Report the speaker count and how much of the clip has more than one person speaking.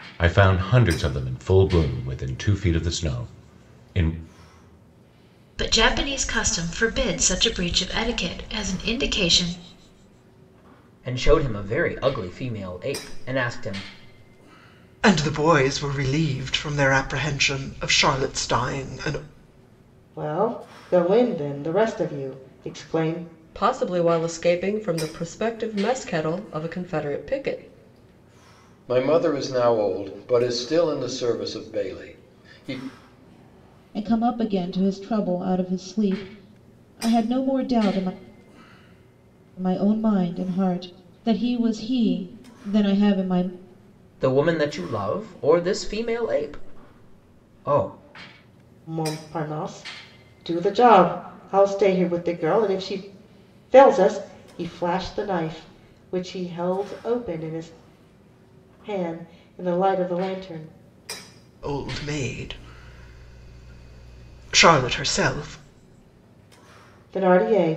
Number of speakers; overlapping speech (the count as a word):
eight, no overlap